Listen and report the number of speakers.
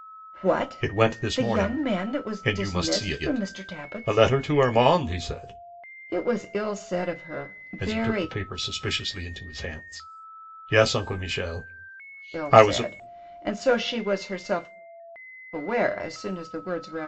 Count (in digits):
2